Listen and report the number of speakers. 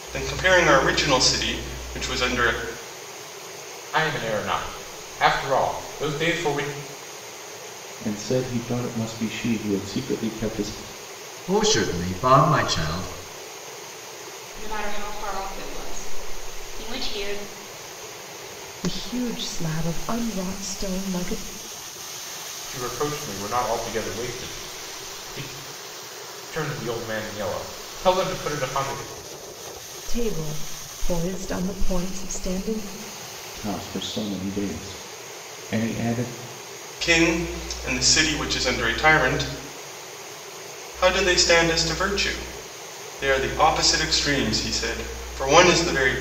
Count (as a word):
six